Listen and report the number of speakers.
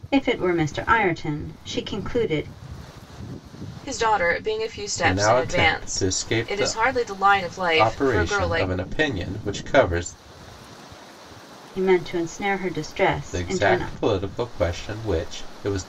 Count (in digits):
3